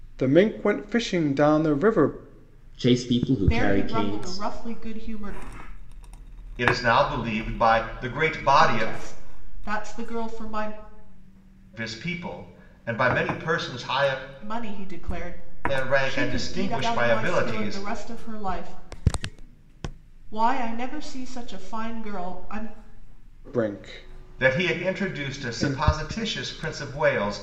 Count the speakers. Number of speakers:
four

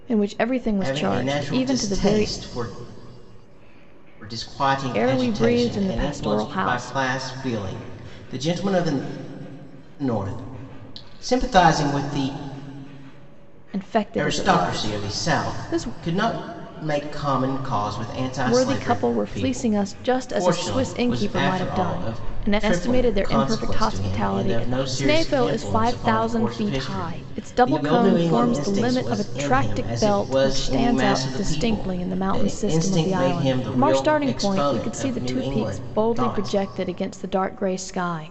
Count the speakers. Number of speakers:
two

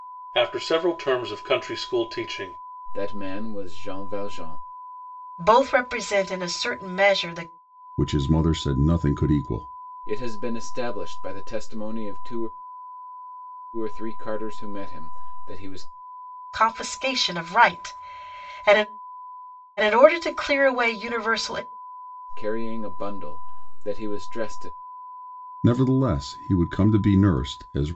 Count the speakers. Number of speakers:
four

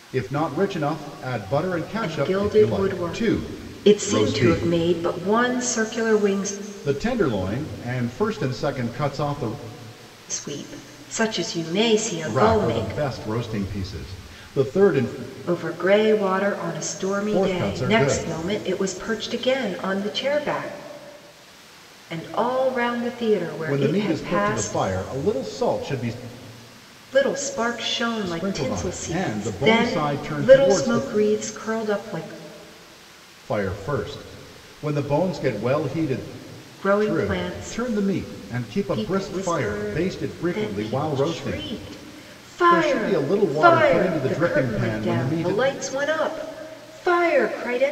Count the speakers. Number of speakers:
two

